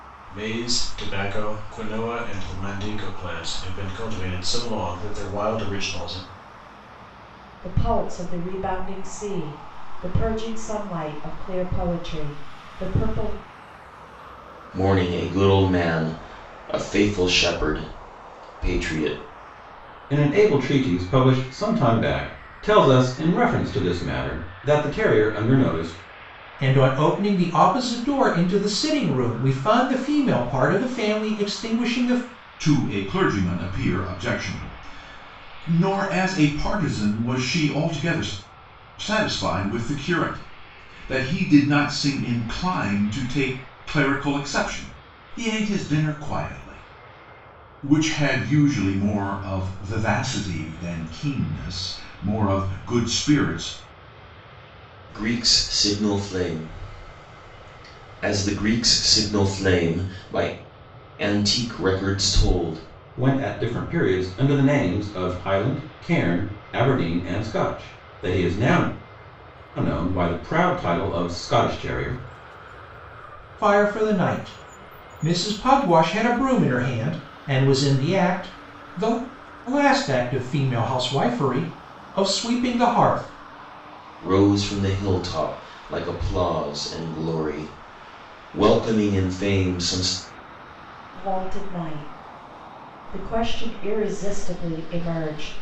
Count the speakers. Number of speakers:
six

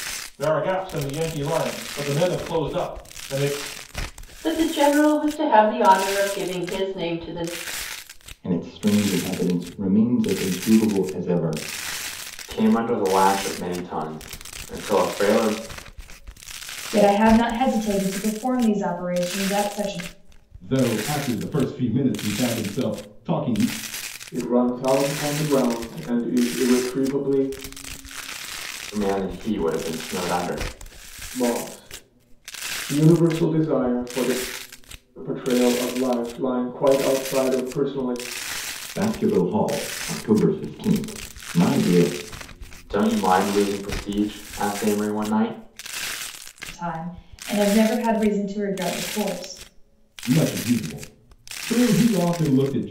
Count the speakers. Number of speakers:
seven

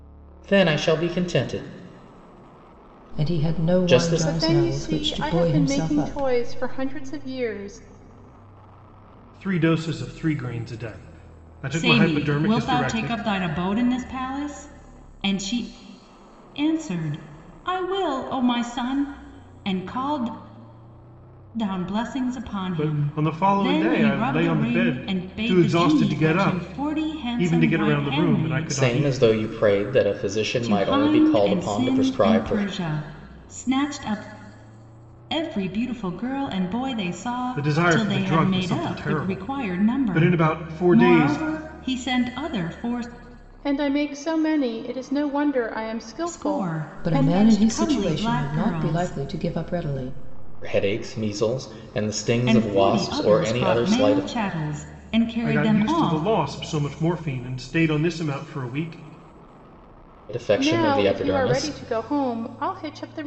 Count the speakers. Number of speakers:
five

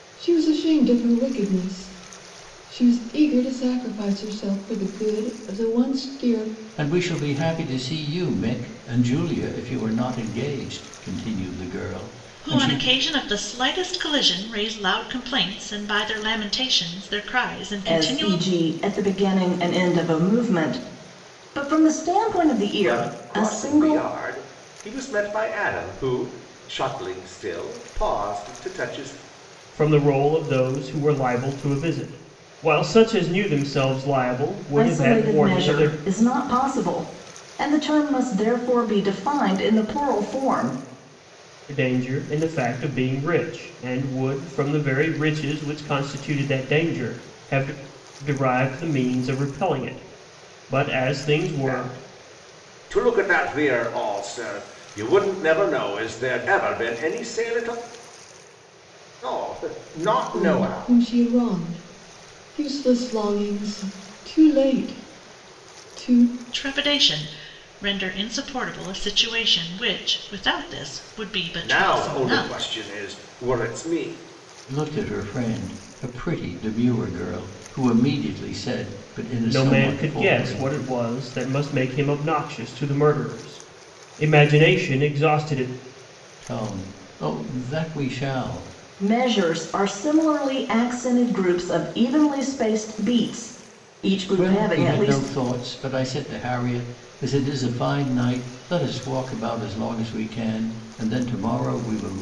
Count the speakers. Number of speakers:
six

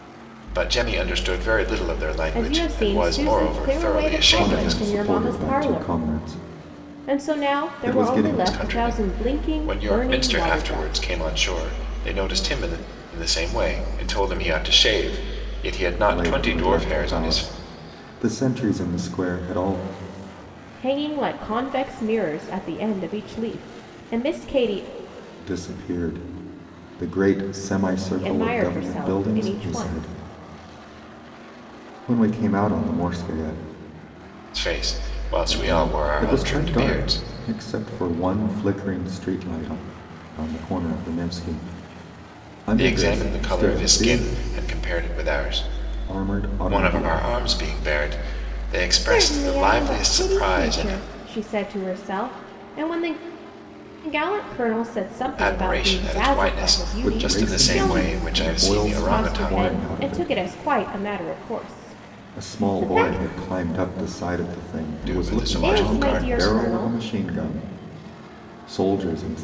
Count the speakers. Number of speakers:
three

